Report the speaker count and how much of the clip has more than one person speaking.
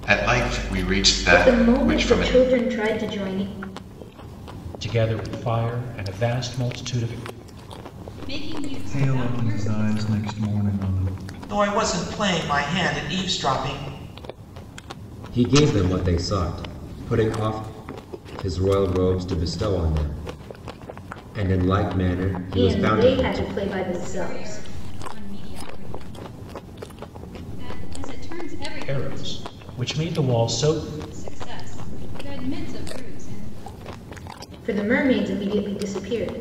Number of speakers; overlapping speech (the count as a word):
seven, about 12%